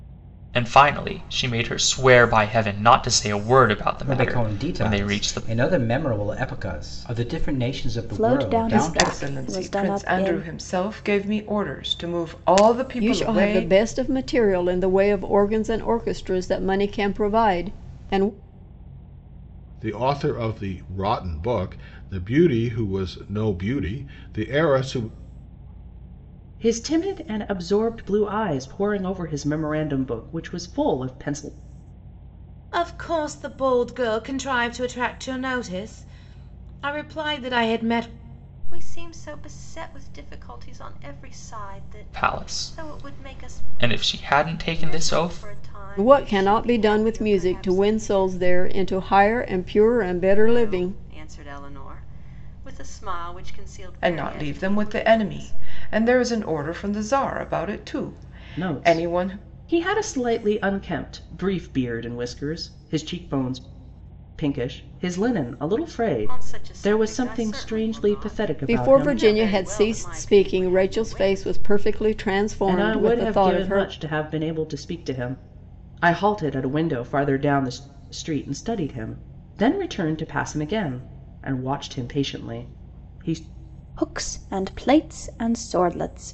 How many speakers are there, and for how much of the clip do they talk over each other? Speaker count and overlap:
9, about 22%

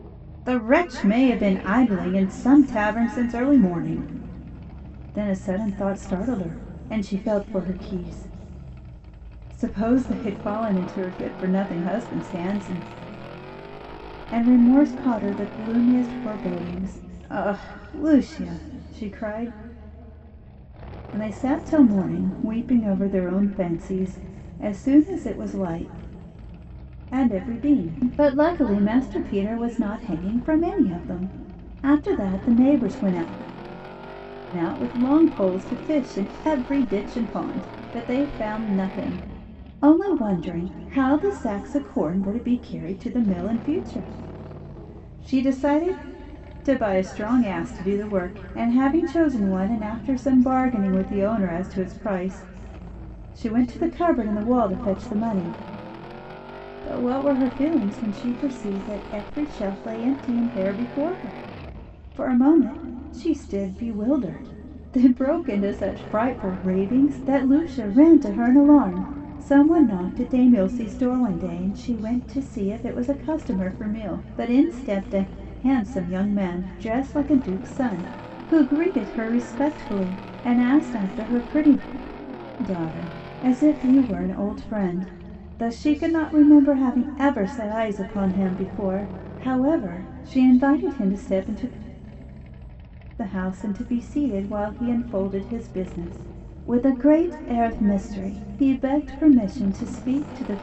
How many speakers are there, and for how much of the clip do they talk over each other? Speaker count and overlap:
1, no overlap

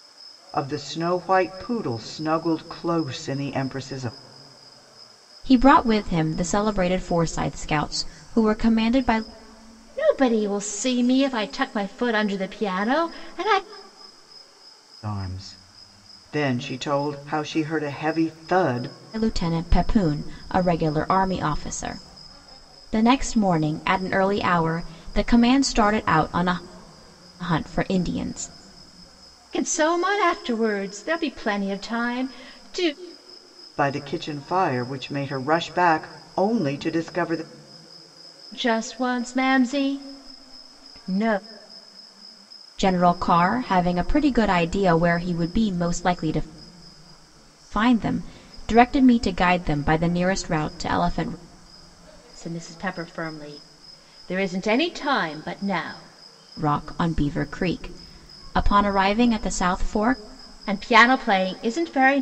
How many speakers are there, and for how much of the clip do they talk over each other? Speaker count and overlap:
3, no overlap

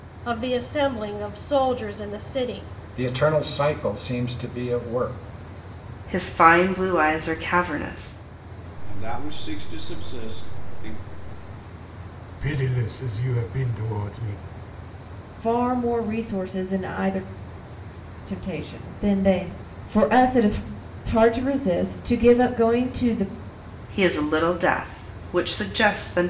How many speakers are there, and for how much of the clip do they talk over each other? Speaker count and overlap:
6, no overlap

